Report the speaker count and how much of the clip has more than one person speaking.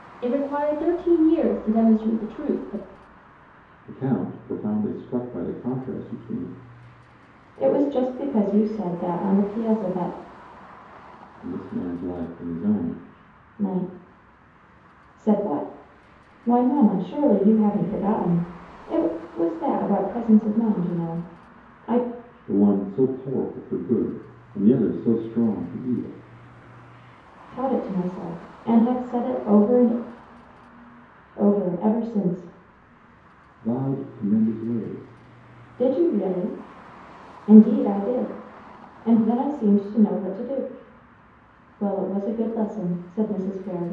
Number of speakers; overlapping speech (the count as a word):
three, no overlap